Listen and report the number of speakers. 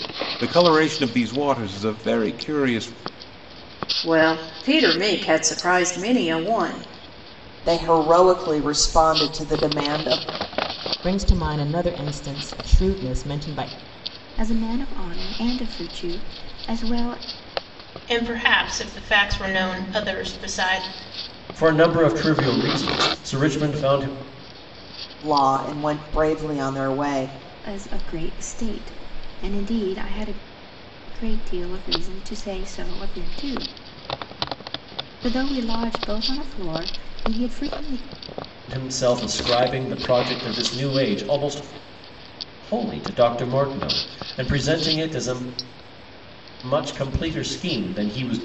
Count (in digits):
7